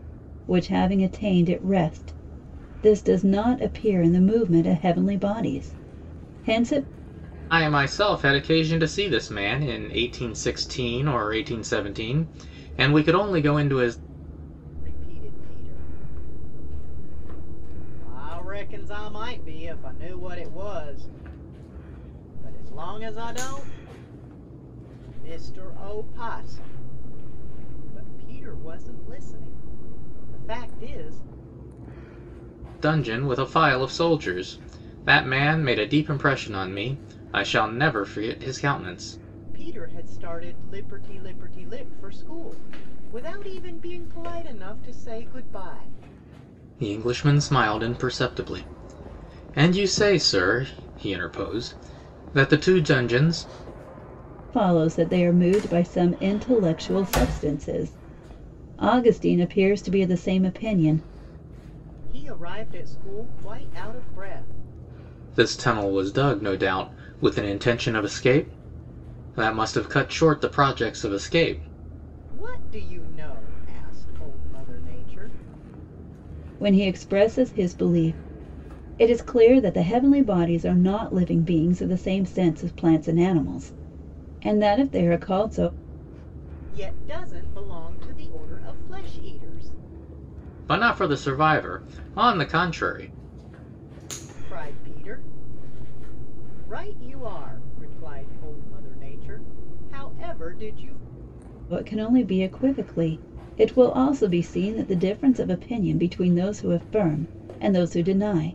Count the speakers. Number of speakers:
three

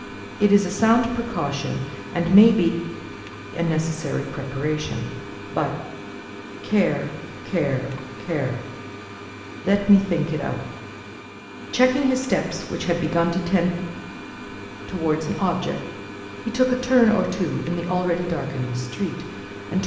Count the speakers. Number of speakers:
one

